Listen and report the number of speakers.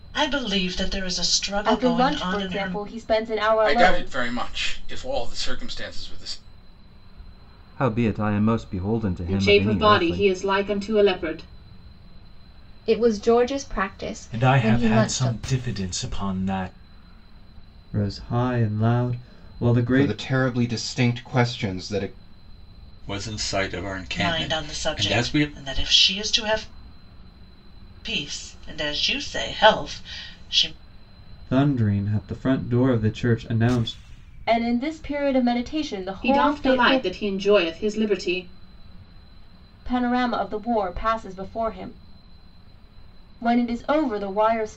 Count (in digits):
10